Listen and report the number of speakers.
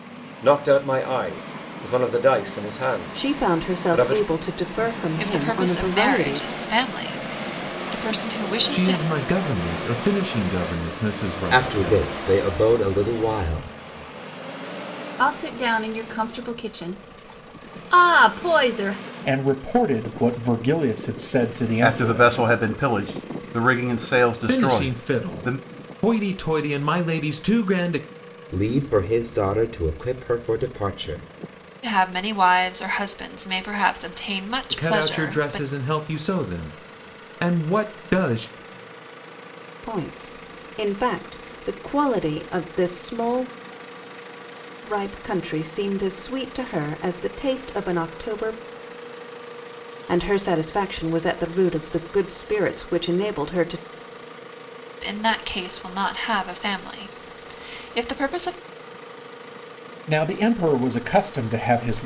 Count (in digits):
8